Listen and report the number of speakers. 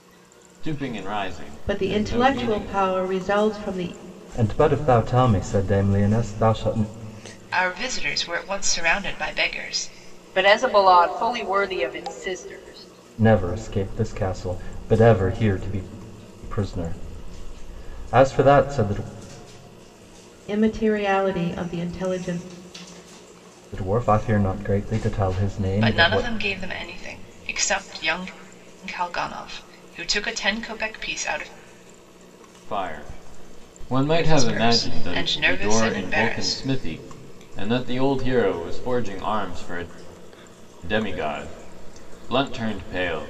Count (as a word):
five